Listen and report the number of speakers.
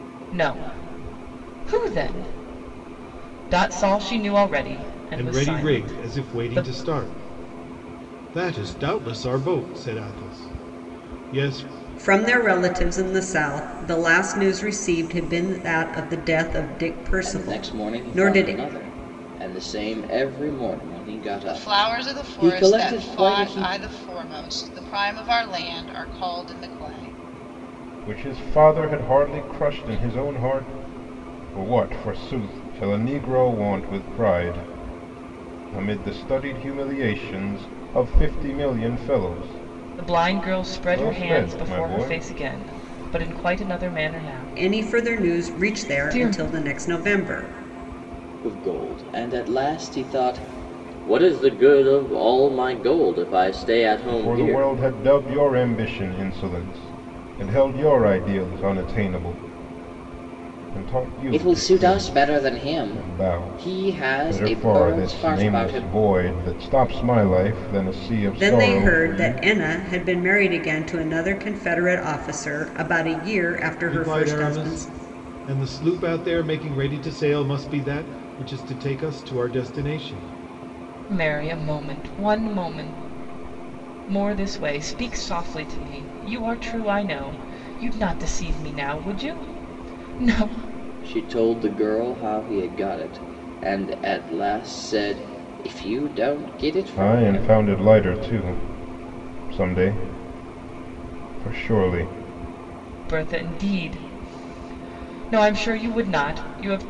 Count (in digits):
6